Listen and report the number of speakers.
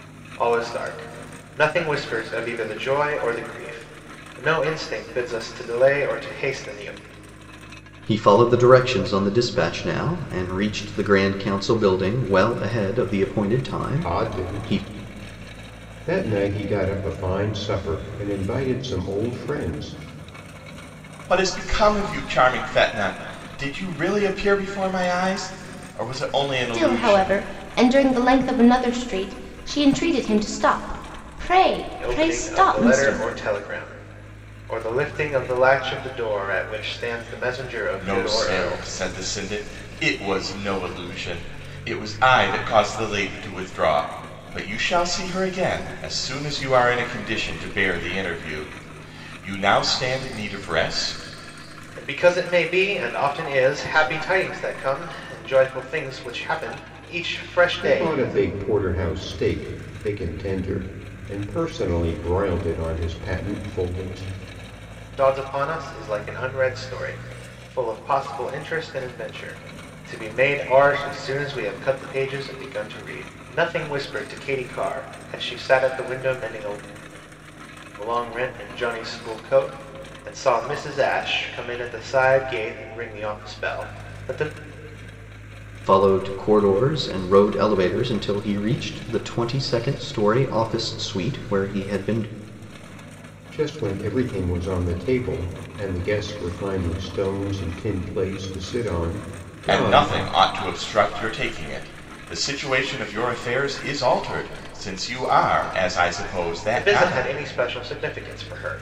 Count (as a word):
five